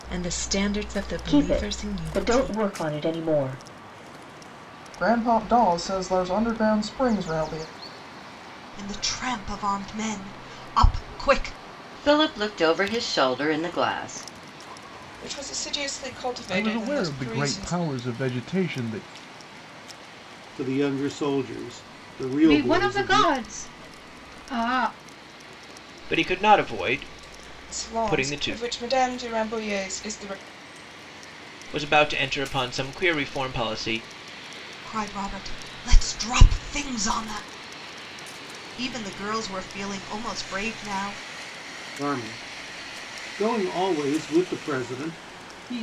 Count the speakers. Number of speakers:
10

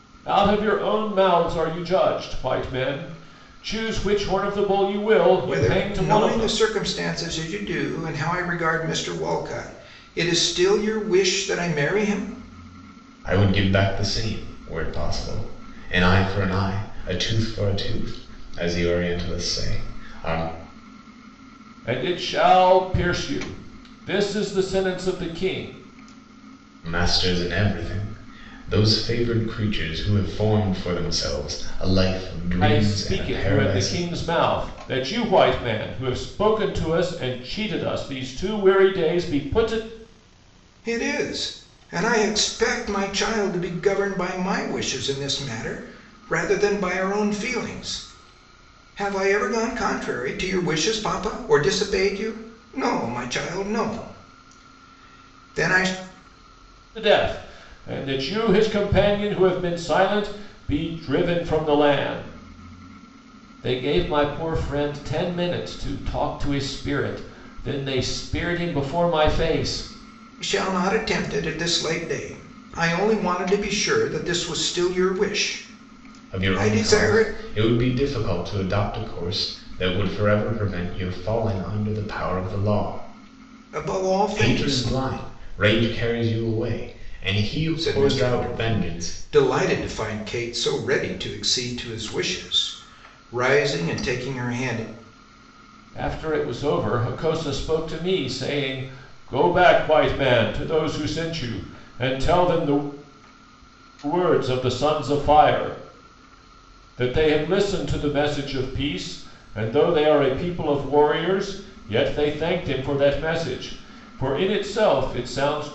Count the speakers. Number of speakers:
3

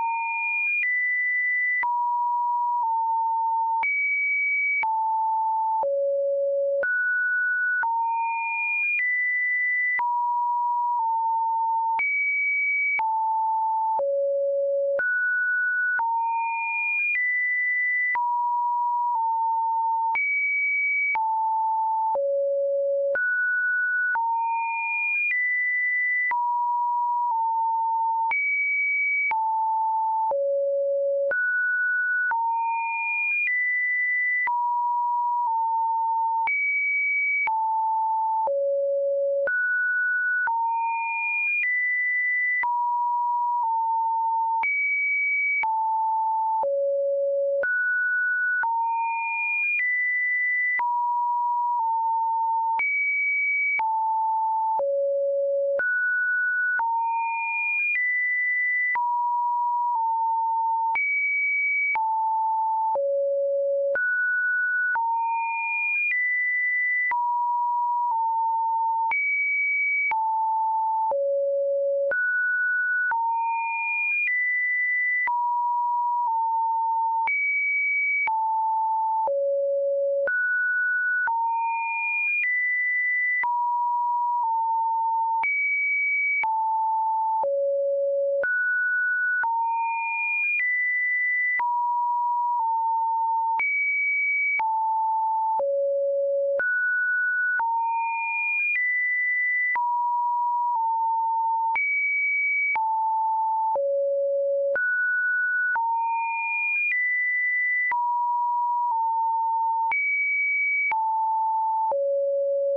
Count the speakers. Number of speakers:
0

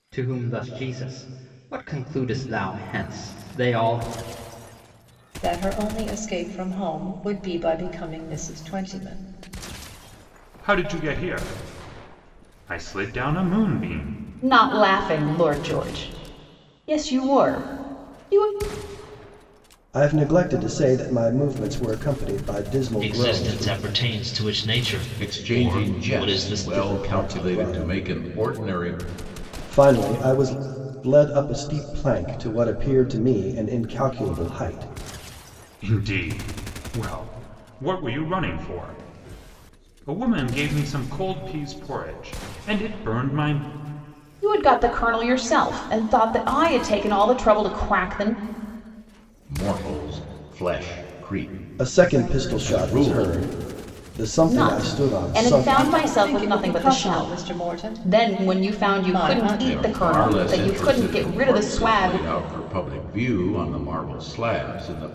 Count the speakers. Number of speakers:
7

